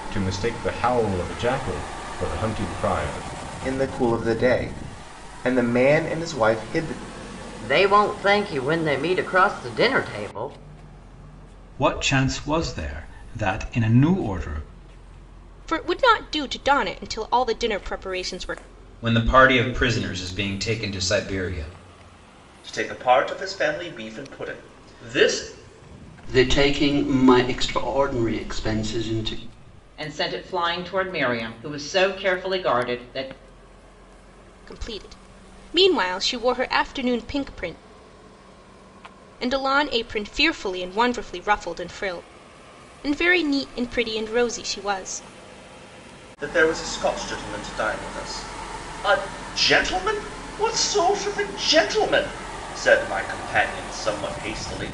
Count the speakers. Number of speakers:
nine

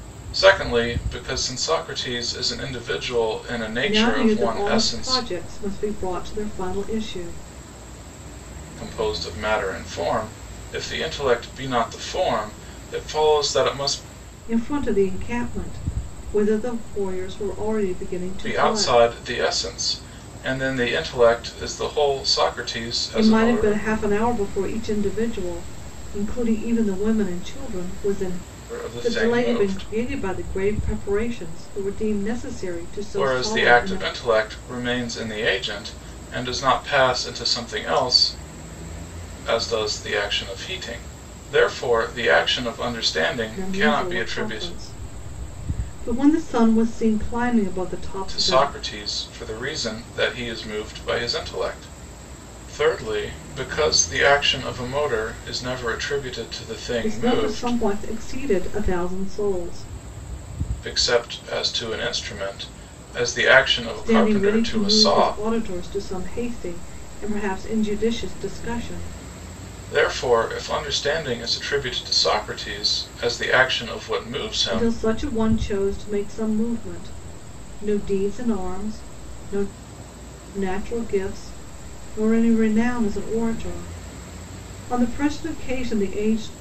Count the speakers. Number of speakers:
two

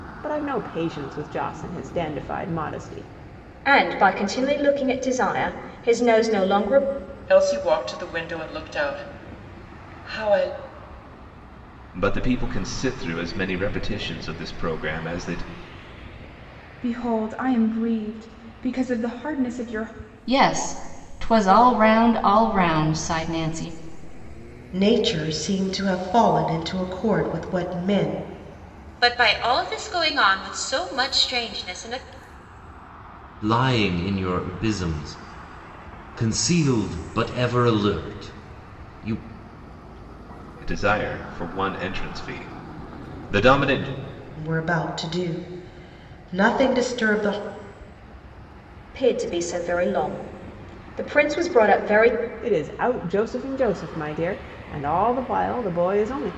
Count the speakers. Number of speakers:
nine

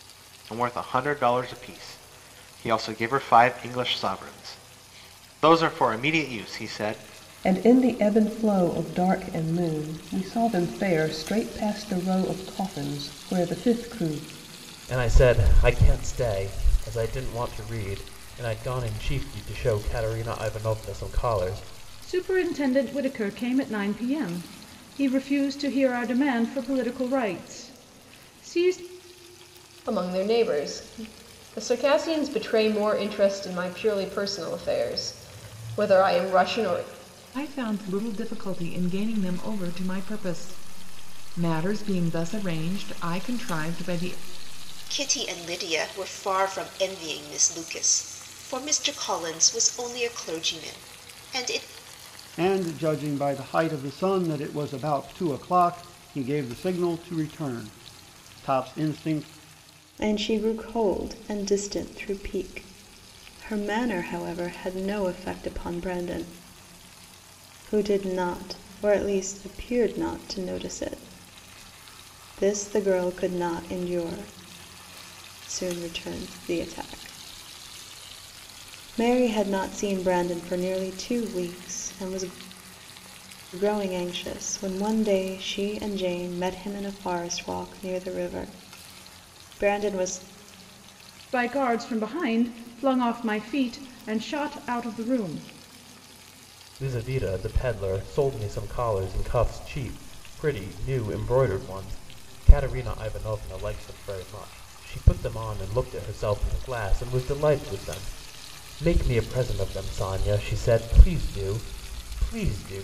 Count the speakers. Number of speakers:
nine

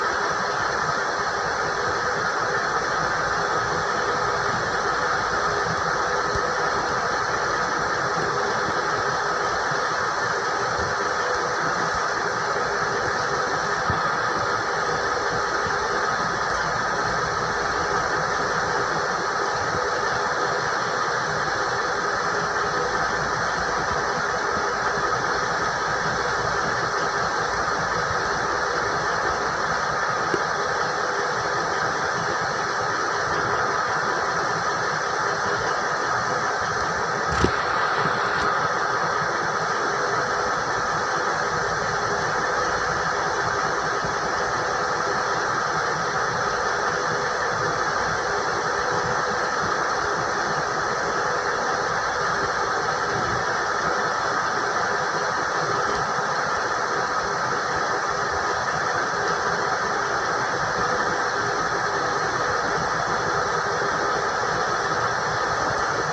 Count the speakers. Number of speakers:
zero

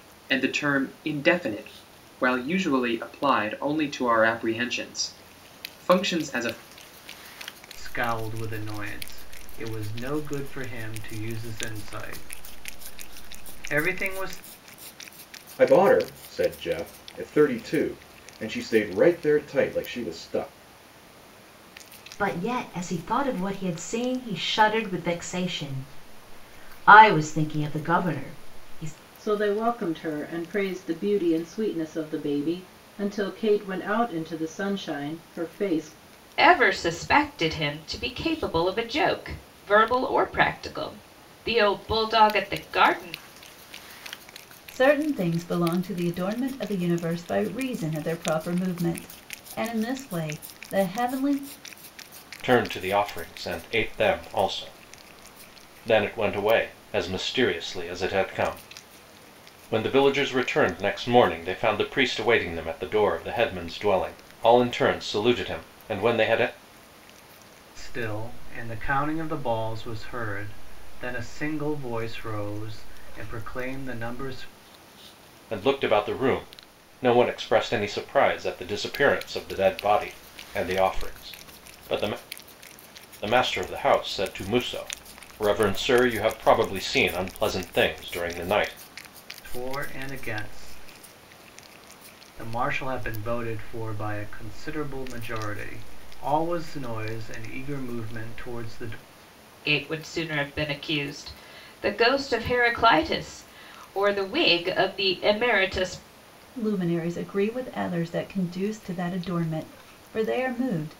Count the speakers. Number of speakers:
eight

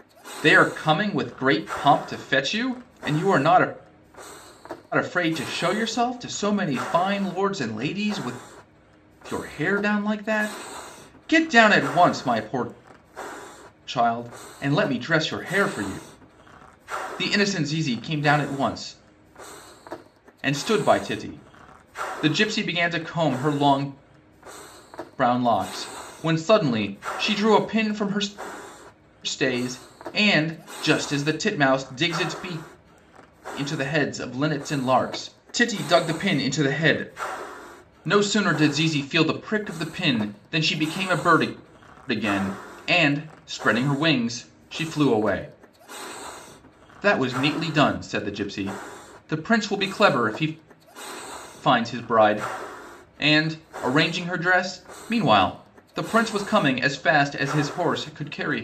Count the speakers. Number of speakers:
one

